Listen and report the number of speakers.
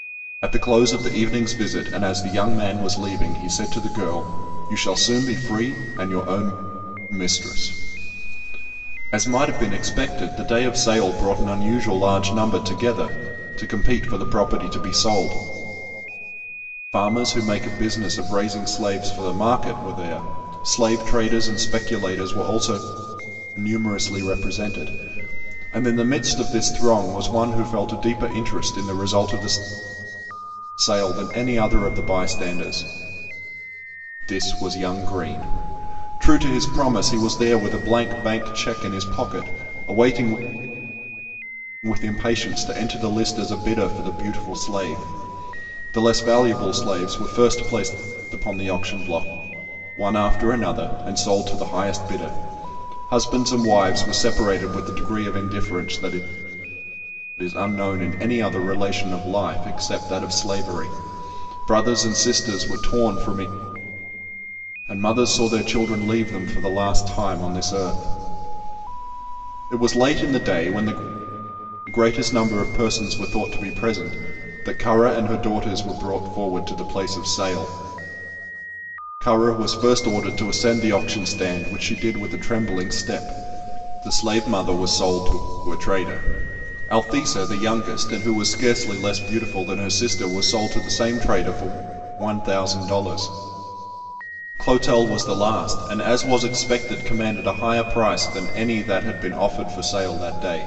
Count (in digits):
1